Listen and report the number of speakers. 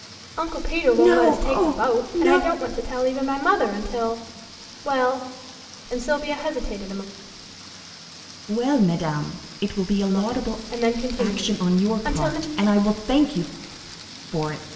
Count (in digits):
2